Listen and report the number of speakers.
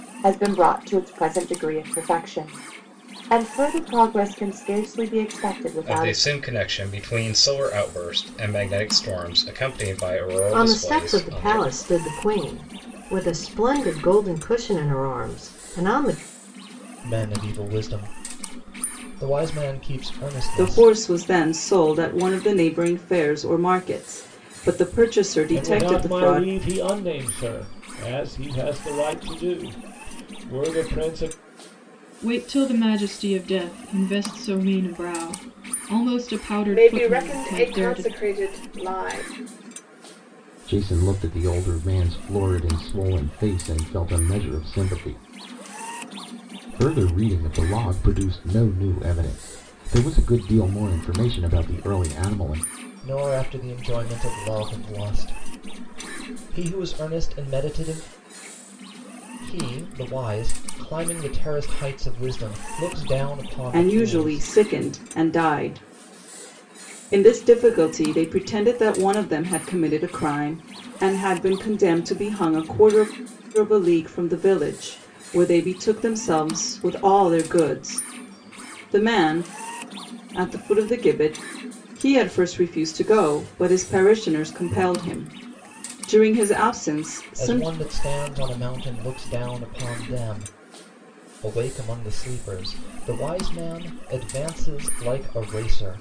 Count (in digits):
9